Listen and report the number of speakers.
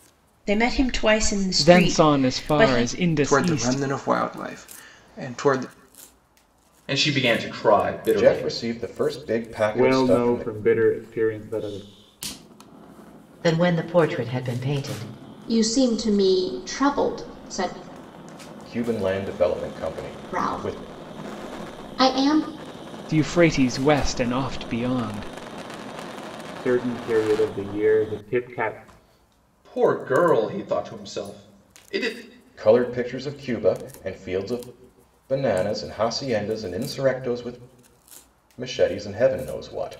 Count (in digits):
8